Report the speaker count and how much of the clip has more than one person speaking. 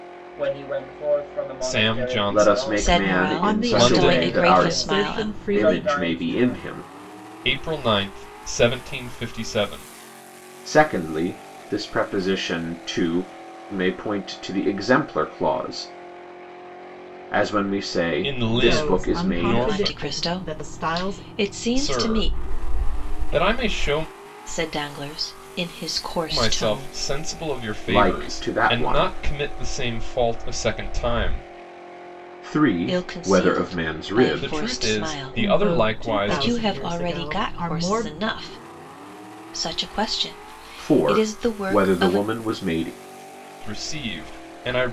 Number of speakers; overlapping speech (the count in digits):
5, about 38%